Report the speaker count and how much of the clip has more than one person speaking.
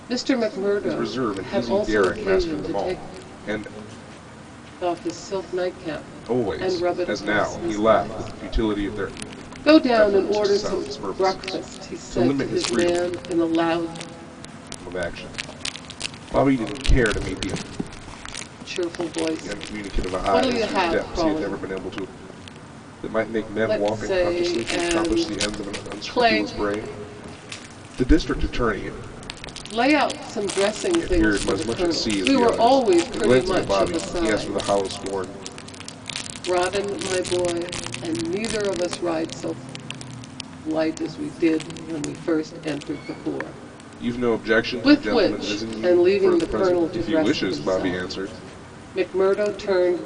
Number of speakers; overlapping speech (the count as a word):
two, about 41%